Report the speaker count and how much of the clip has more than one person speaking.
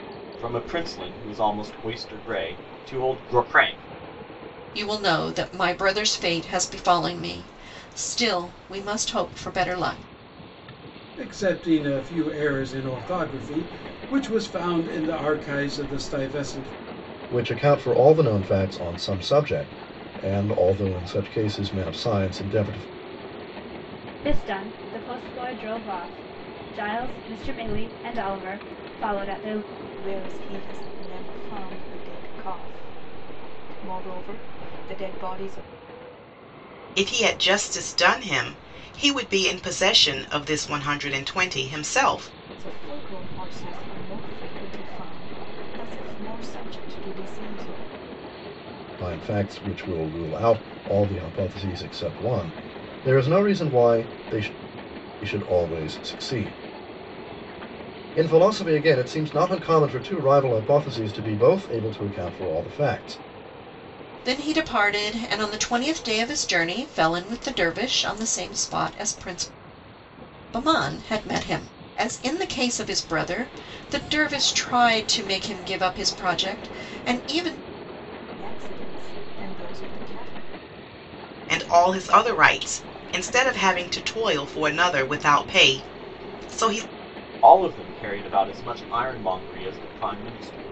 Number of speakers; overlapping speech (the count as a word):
seven, no overlap